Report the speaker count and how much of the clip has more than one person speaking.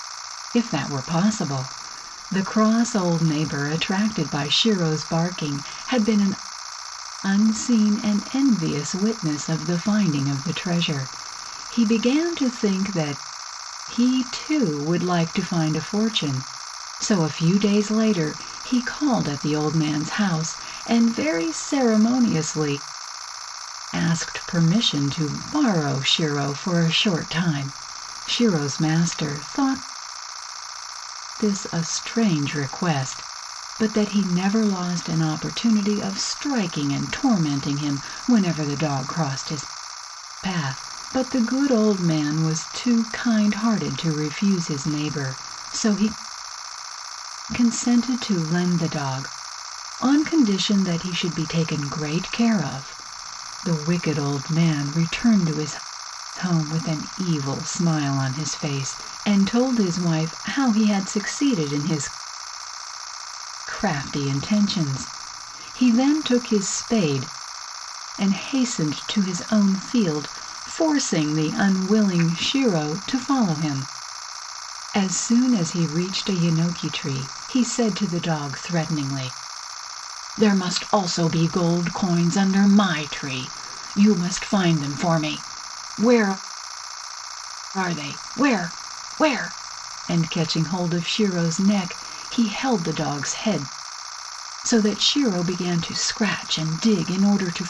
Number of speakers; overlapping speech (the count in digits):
1, no overlap